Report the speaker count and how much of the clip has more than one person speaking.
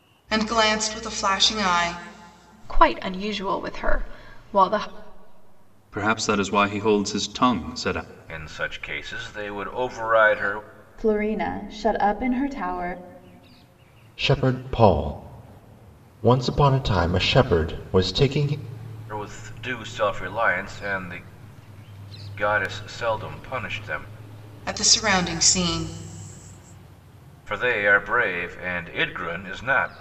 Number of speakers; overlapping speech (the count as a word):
six, no overlap